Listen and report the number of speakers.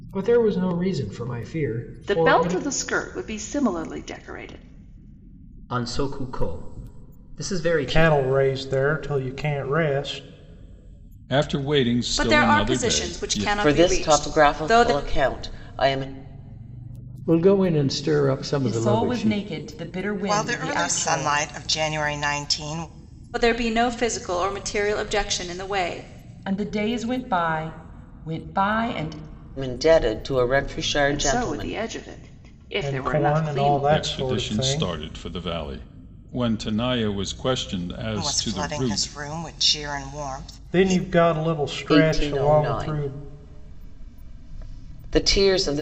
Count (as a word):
ten